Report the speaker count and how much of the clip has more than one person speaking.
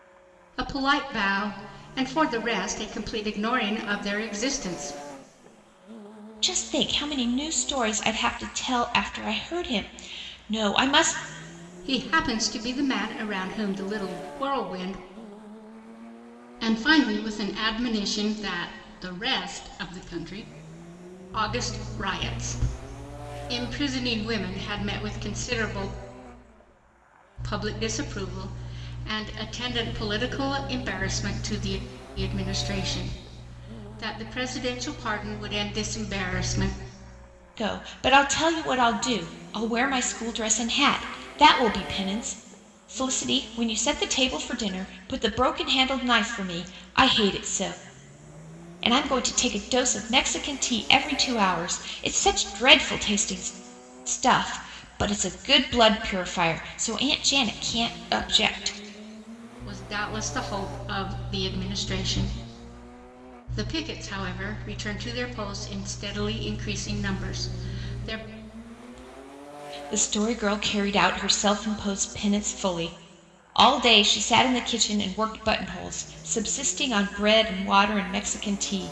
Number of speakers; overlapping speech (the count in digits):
2, no overlap